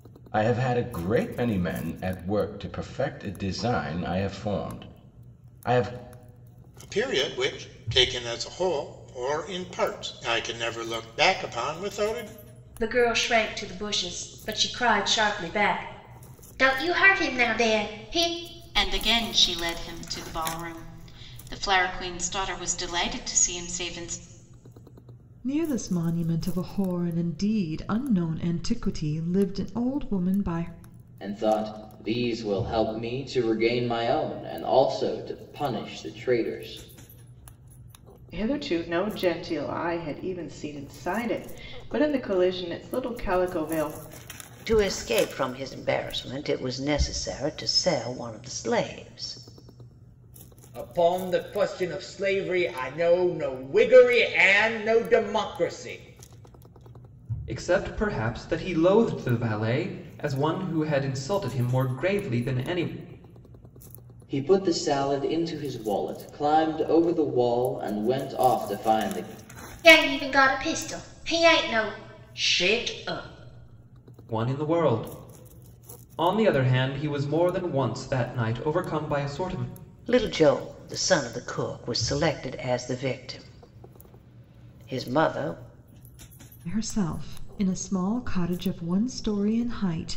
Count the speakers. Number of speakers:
10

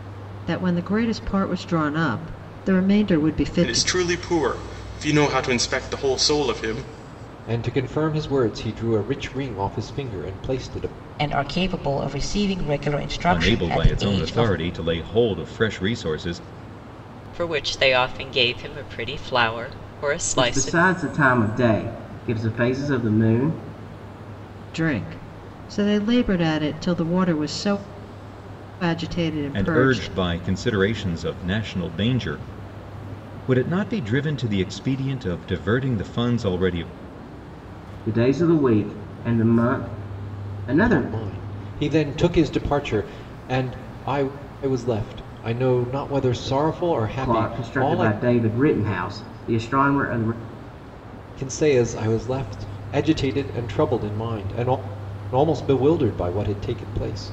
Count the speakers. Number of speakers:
7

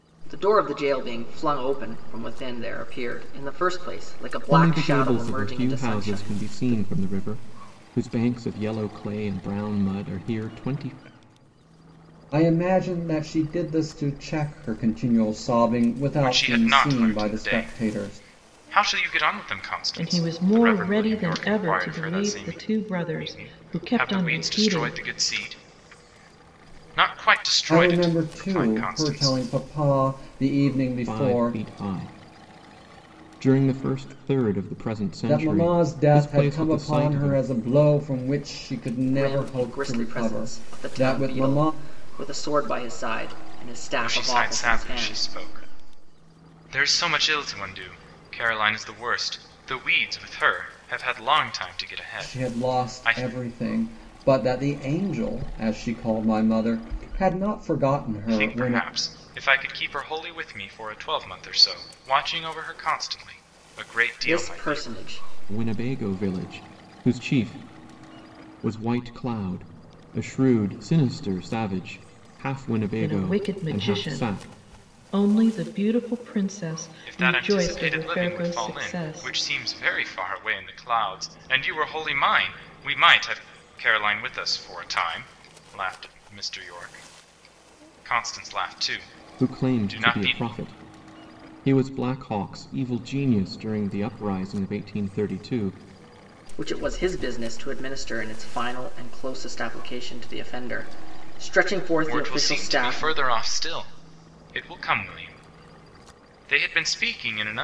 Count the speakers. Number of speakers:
5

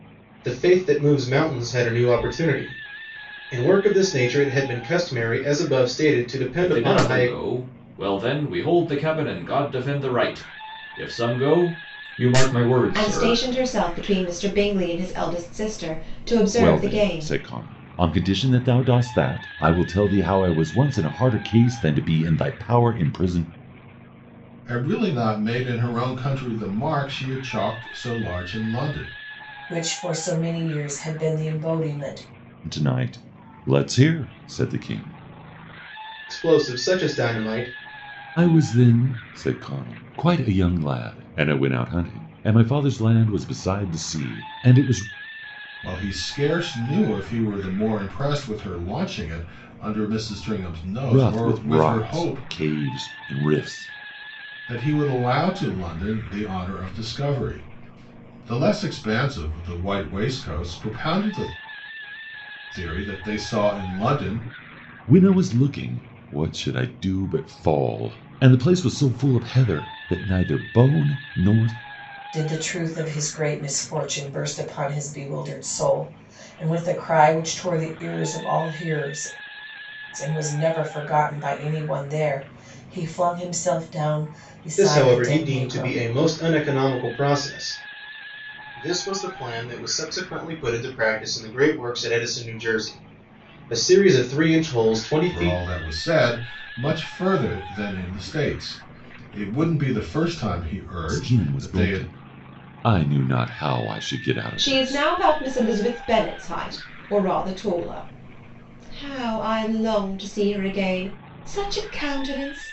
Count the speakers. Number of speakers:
6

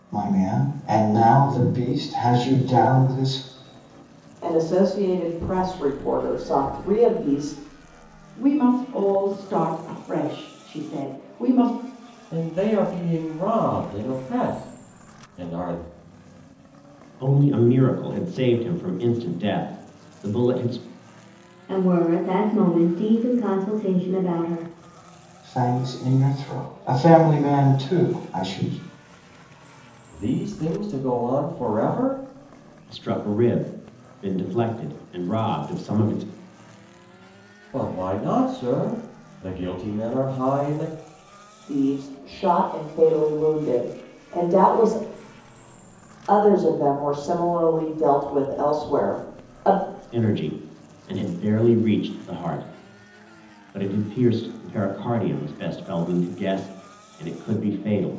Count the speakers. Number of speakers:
6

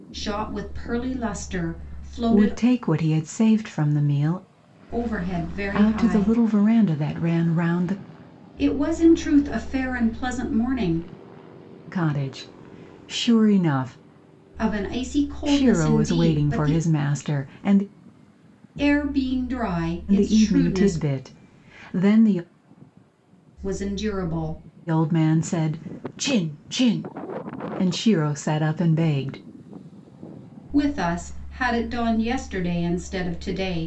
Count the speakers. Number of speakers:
2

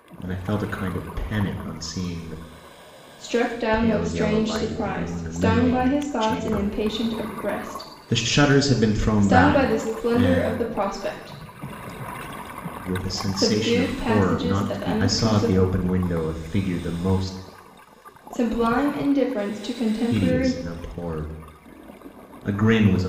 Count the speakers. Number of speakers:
2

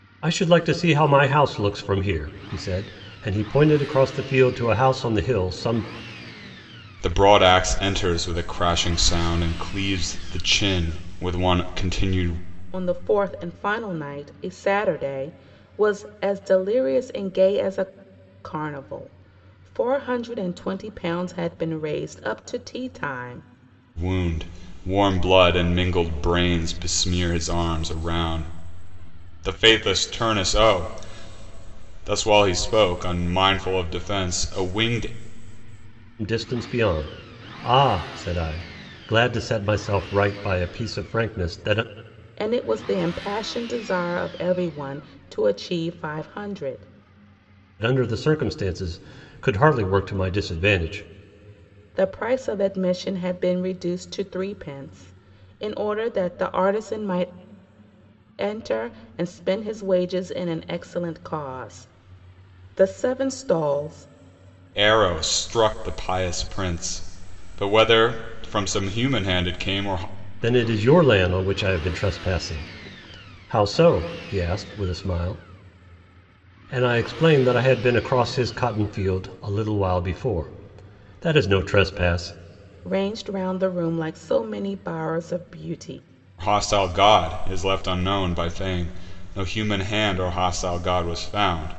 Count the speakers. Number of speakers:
3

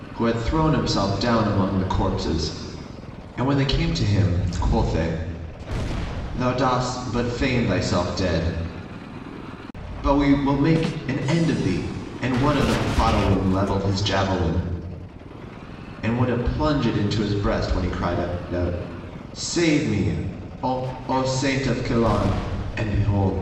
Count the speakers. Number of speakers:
1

